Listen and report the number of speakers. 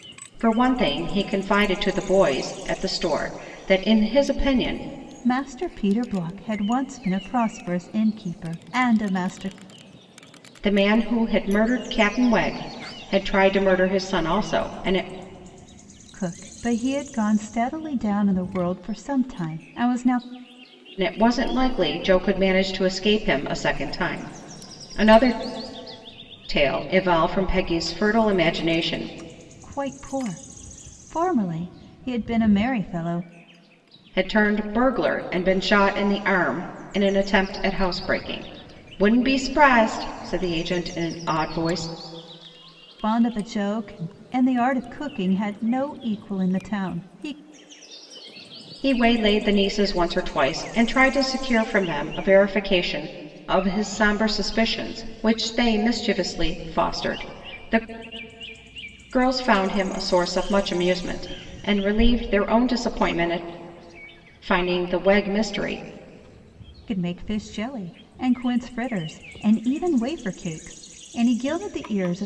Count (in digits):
2